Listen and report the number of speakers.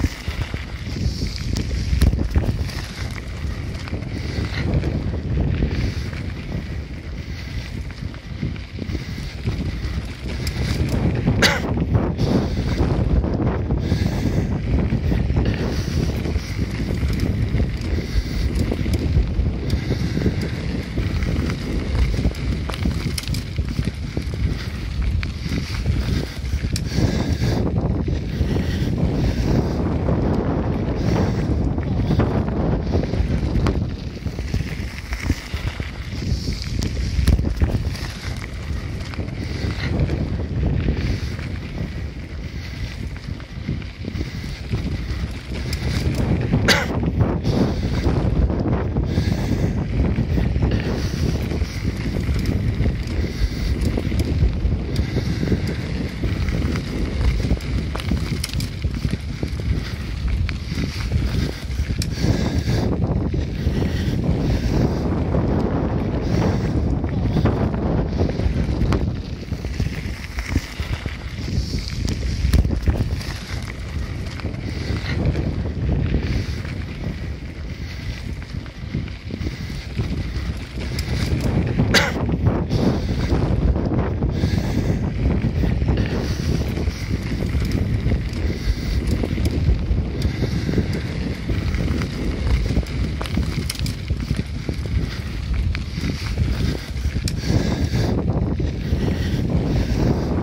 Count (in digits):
0